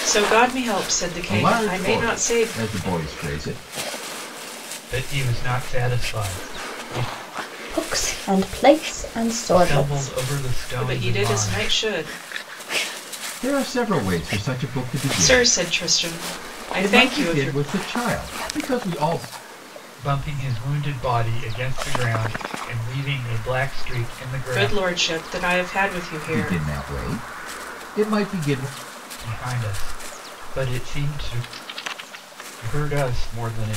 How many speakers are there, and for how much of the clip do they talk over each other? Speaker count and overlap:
four, about 14%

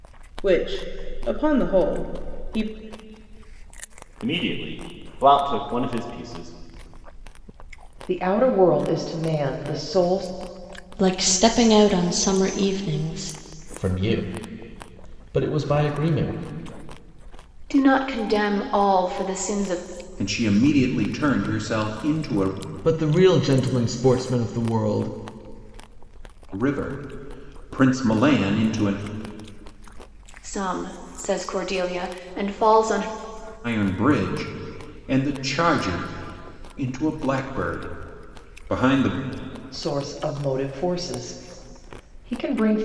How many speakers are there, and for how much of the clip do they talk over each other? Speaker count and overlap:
eight, no overlap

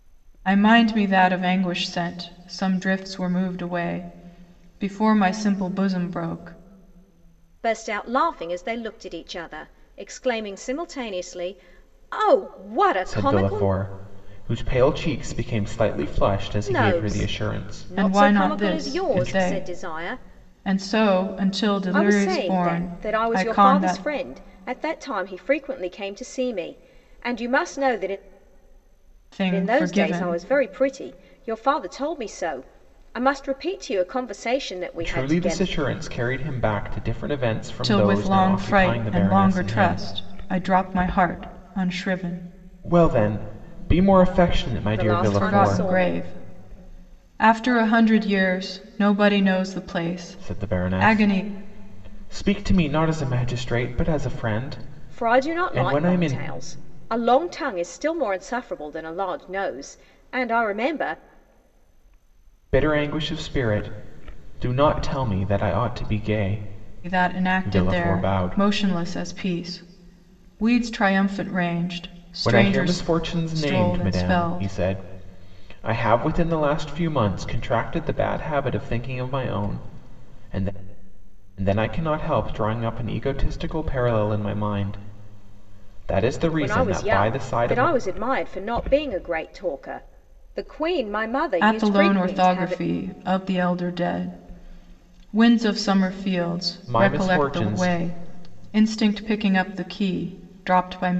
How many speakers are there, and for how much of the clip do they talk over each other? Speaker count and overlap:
three, about 21%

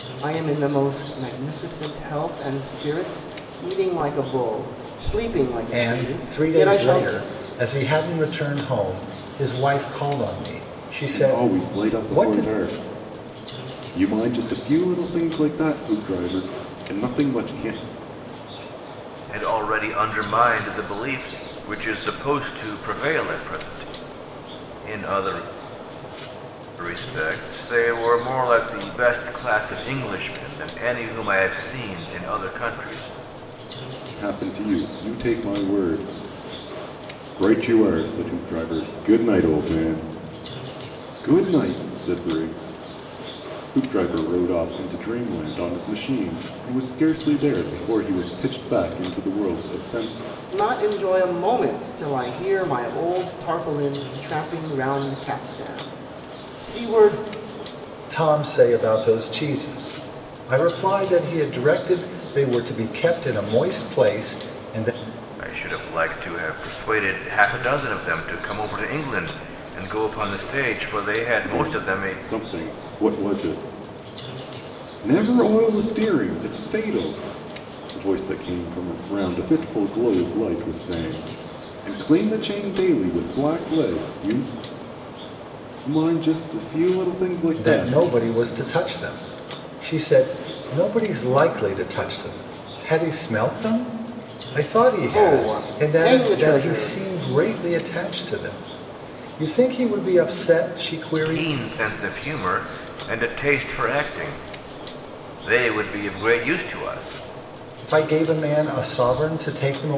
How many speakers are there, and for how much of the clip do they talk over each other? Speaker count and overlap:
four, about 6%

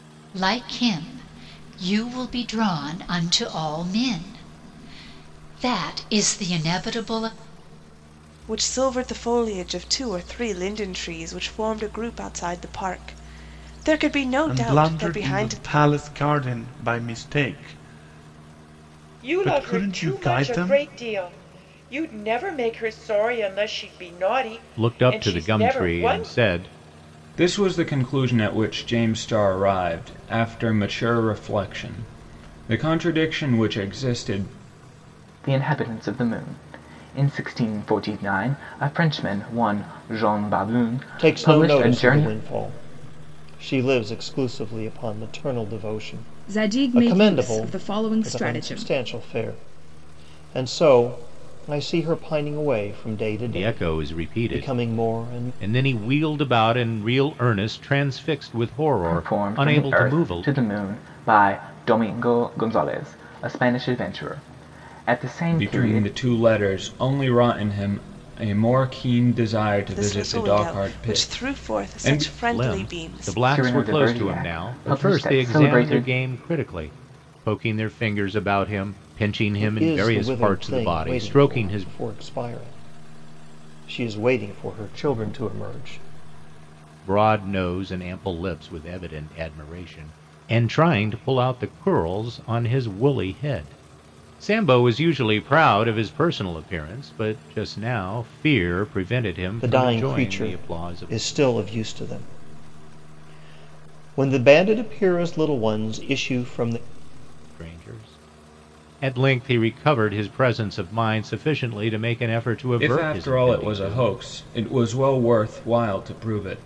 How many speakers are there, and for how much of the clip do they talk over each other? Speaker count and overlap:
nine, about 21%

